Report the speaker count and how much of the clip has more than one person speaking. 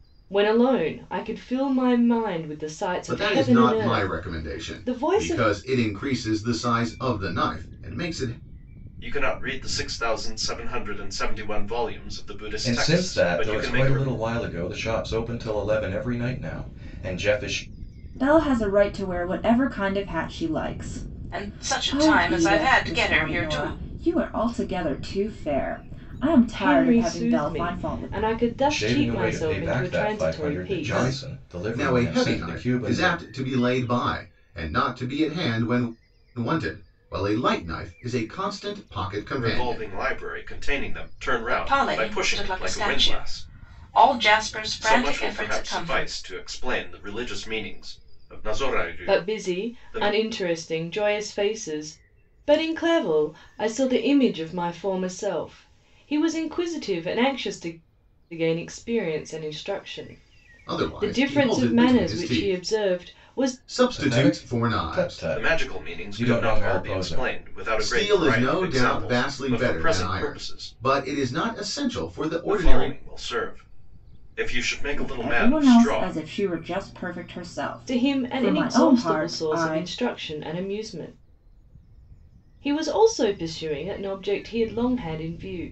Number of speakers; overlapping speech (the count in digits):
6, about 36%